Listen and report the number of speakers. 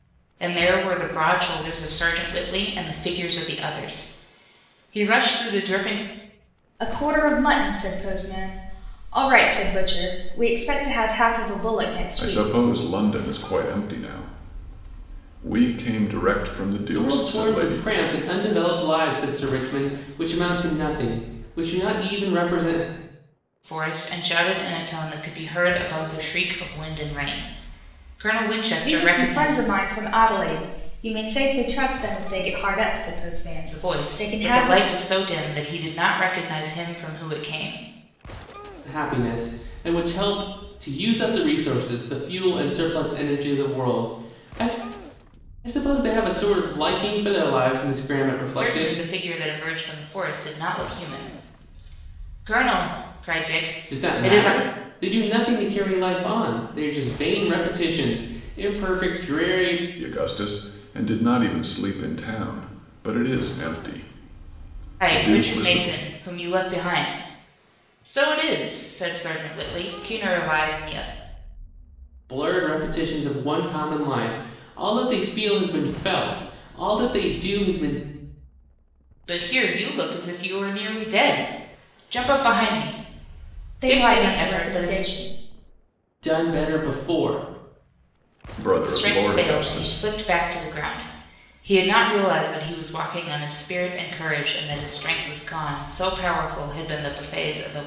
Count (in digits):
4